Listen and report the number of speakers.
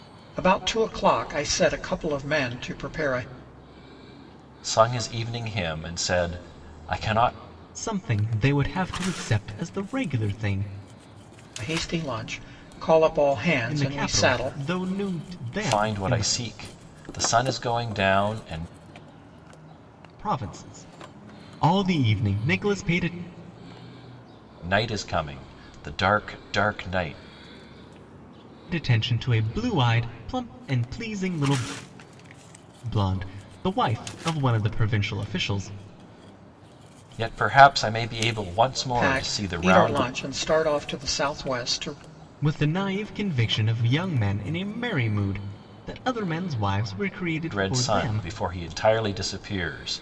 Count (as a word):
three